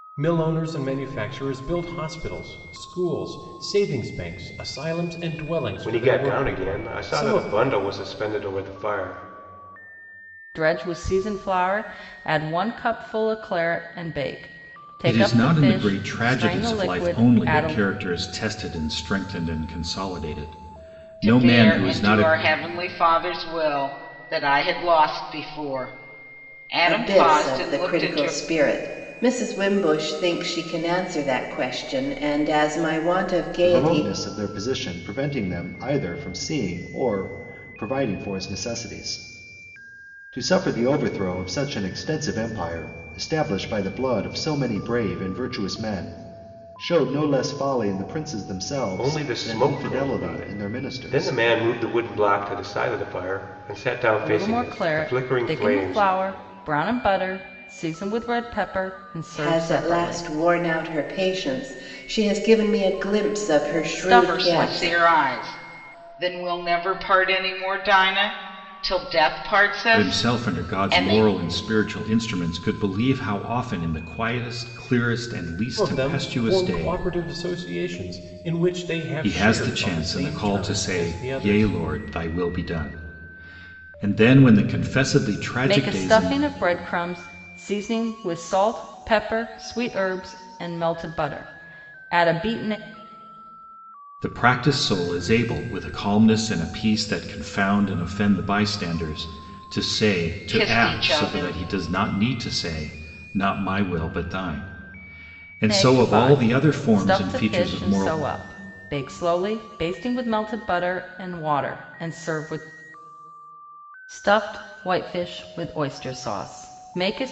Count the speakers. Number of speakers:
seven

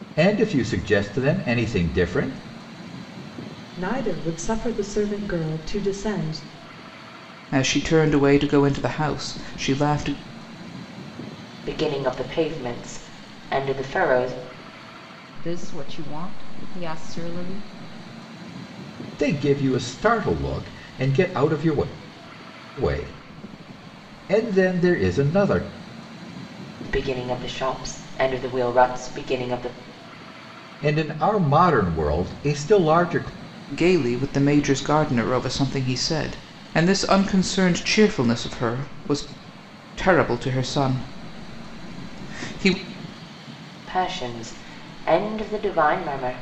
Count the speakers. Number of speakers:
five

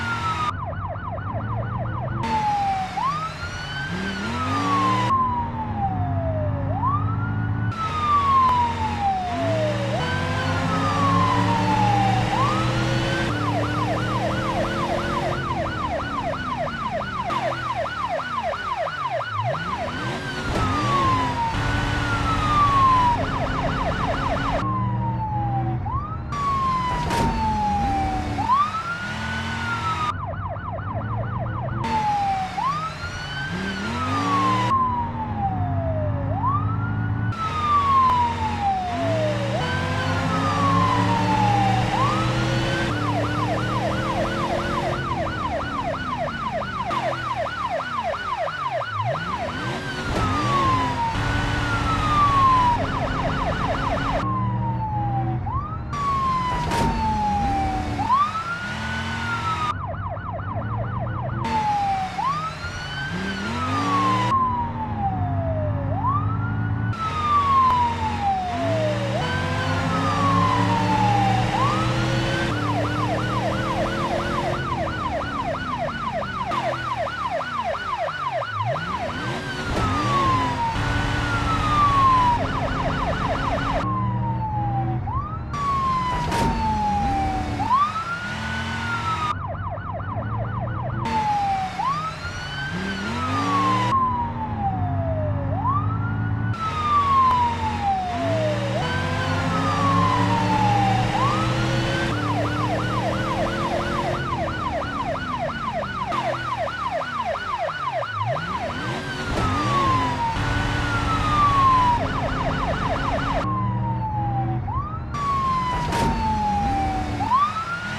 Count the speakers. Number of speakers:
zero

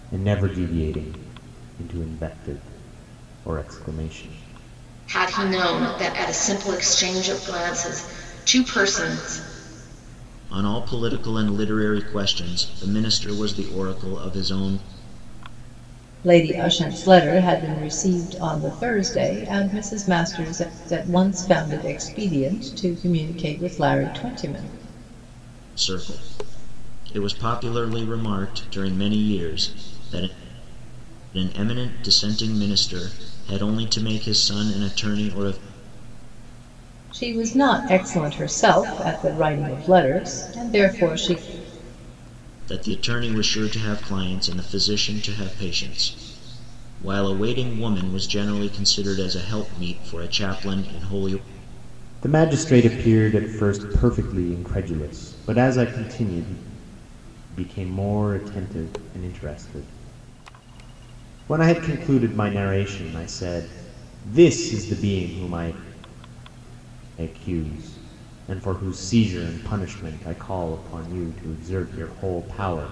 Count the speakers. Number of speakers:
four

